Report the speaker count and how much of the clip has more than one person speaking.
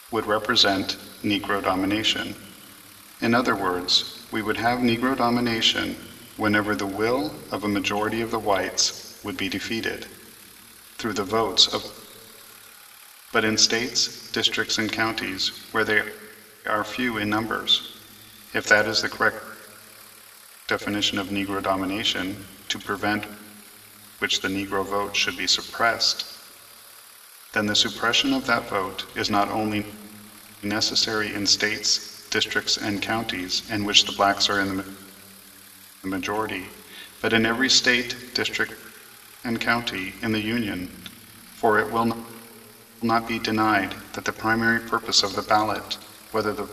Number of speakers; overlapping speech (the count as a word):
one, no overlap